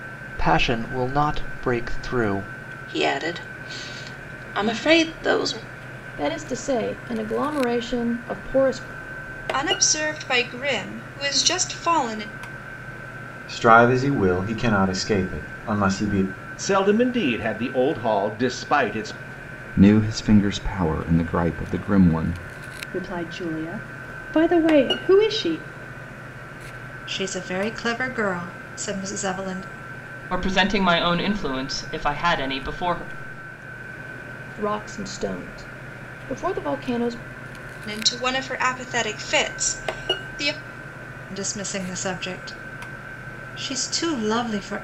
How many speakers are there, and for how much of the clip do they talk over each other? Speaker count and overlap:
10, no overlap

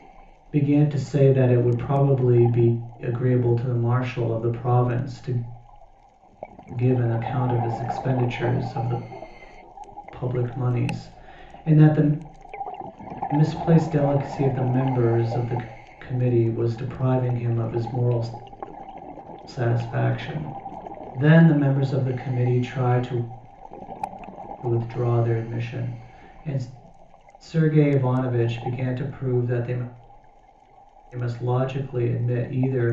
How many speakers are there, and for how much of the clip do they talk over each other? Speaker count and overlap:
1, no overlap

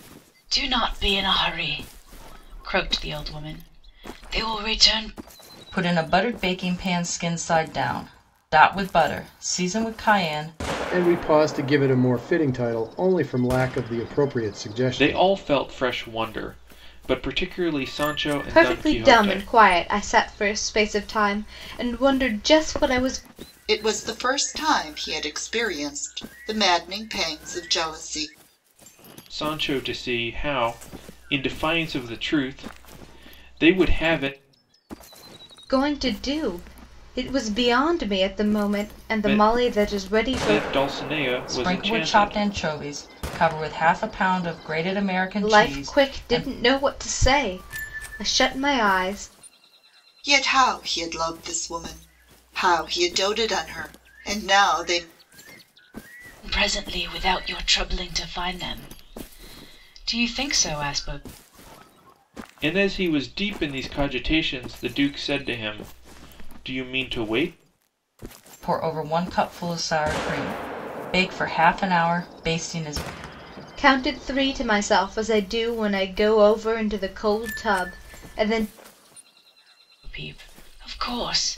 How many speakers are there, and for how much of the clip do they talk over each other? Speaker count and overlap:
6, about 6%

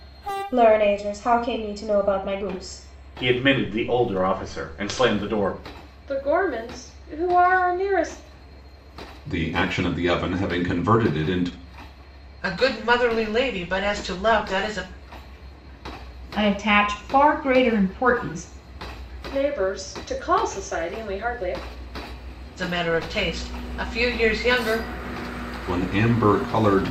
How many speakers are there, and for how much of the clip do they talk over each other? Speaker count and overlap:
6, no overlap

